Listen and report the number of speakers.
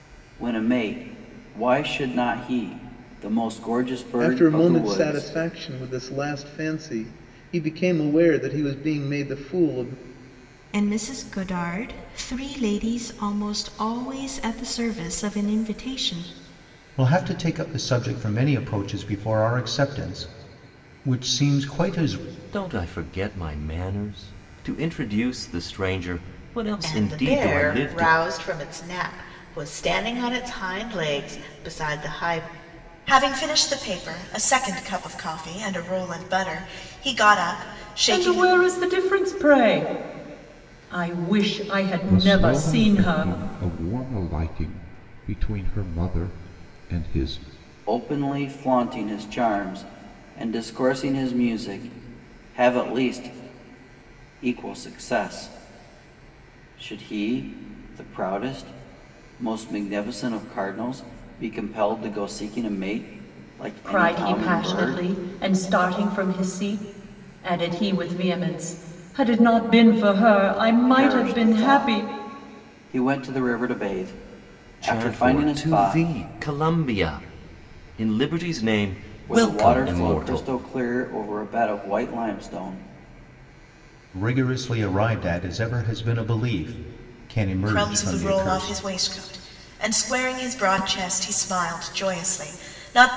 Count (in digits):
9